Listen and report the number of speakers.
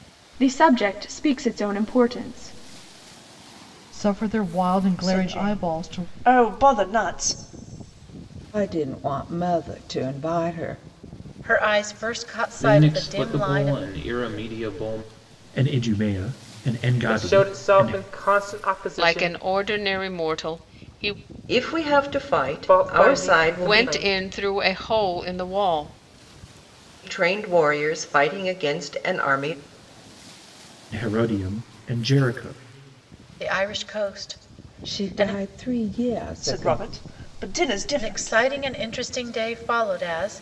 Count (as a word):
ten